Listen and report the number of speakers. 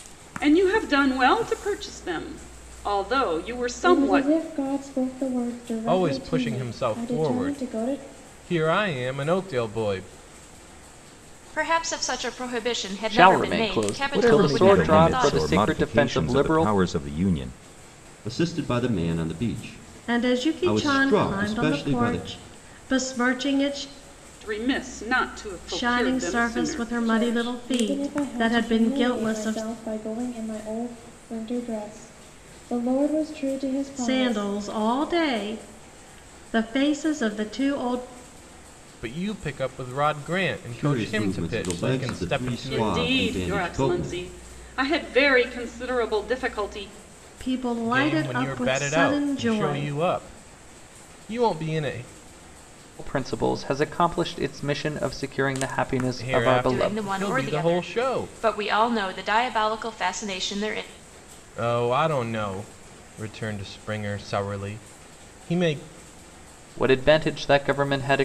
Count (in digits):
8